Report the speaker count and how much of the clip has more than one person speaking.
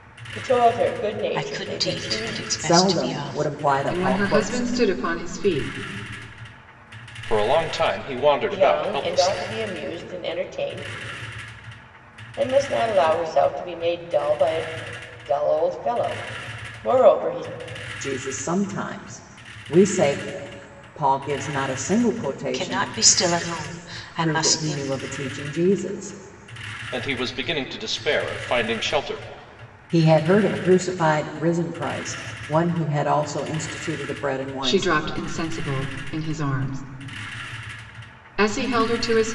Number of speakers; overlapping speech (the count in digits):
5, about 14%